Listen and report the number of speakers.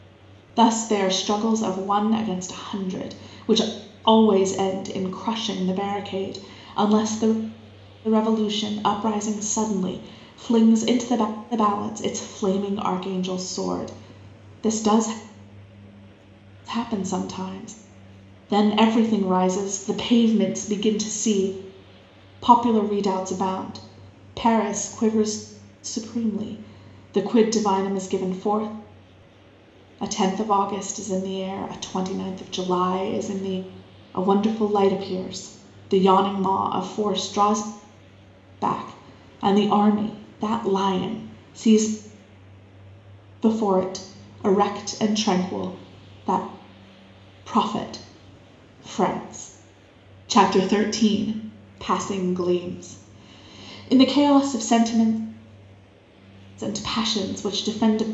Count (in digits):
1